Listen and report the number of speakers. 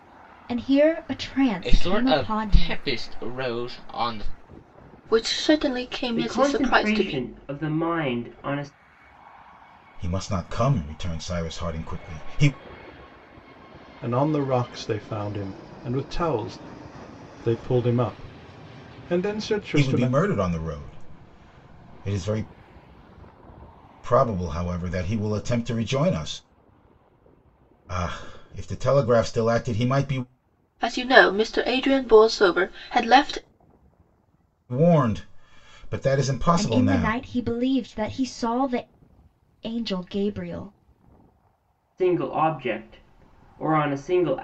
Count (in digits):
6